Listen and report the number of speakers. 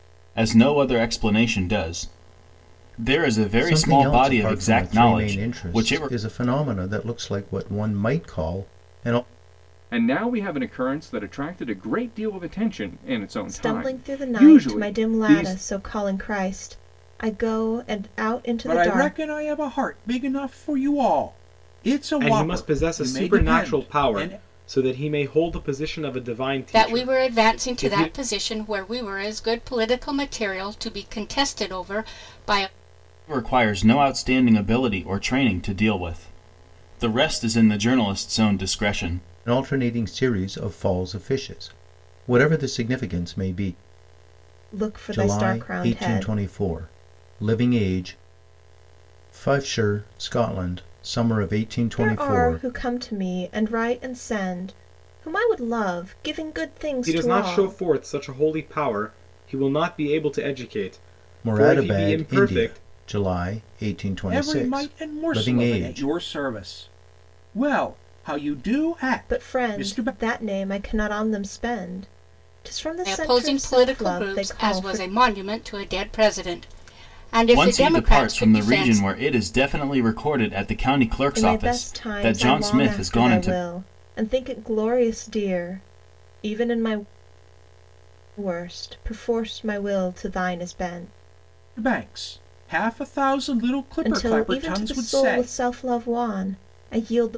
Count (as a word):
seven